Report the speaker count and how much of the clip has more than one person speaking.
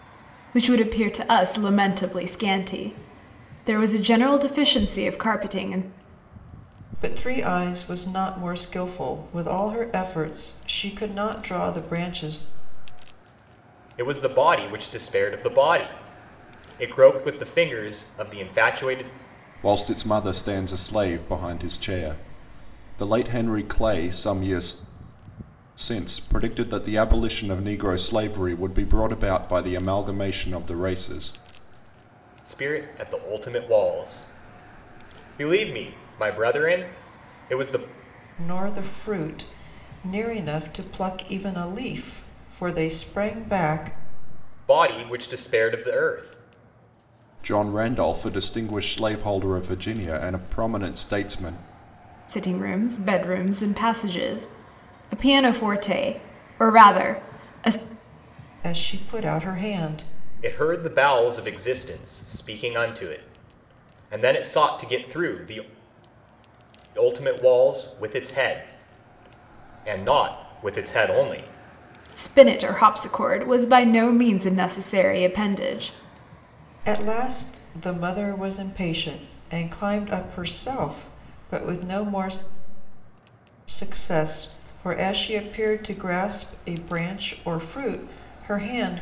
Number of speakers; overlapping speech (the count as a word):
four, no overlap